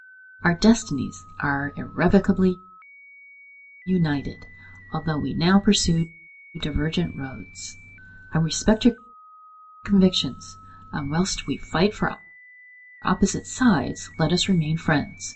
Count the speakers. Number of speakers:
one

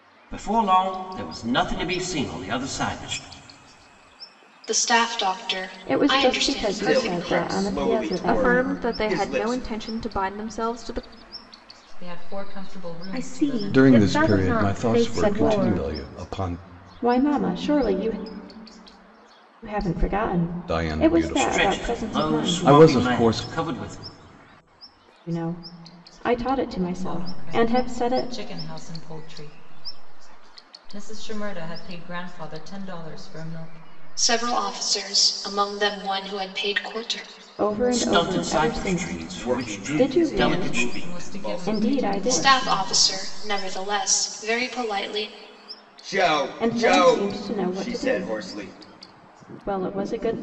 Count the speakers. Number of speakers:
eight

